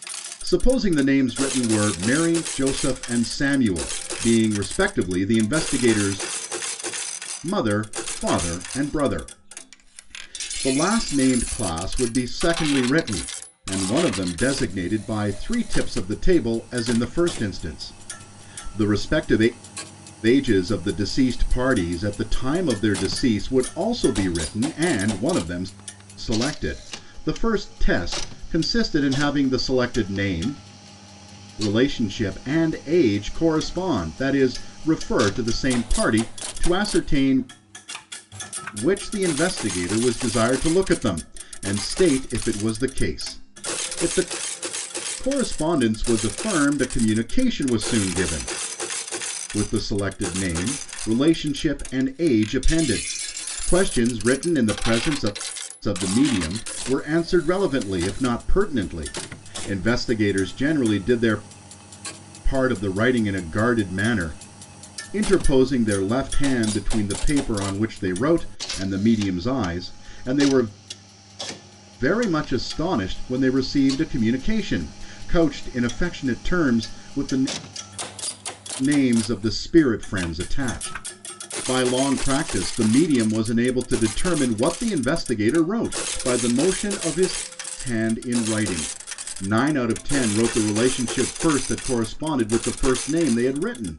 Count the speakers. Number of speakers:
1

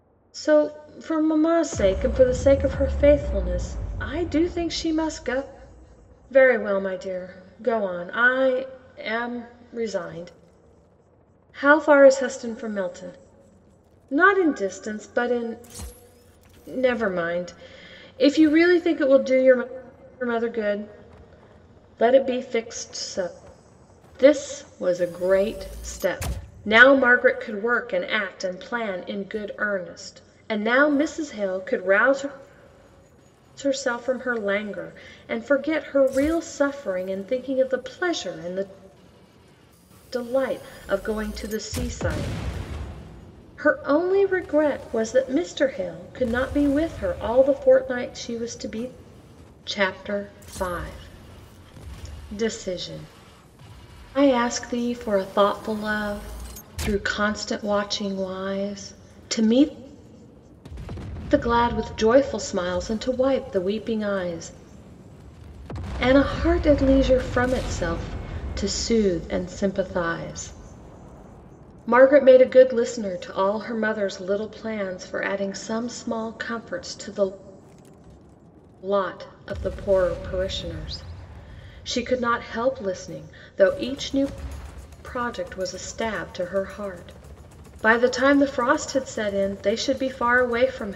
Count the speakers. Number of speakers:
1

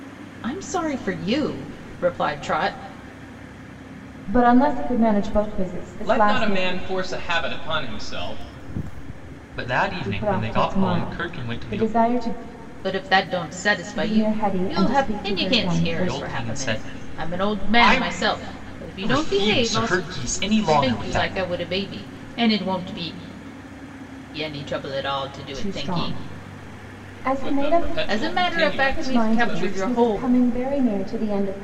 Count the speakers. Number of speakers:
4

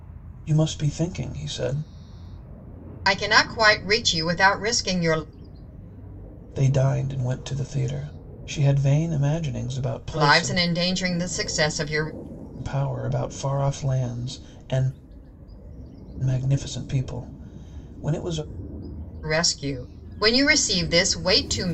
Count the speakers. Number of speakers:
2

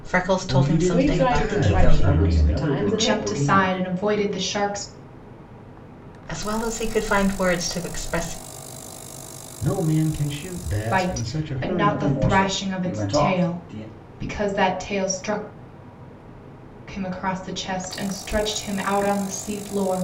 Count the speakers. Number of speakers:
5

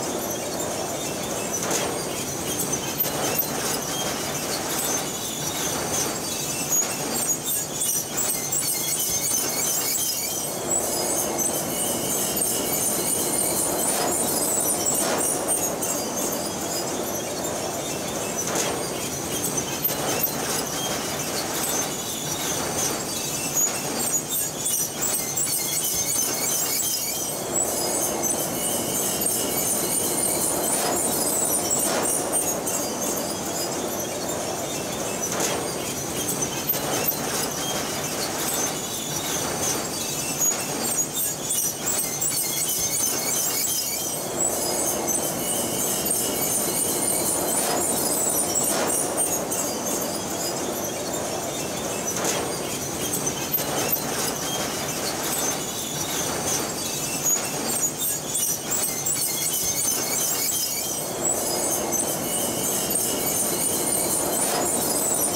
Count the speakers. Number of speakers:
0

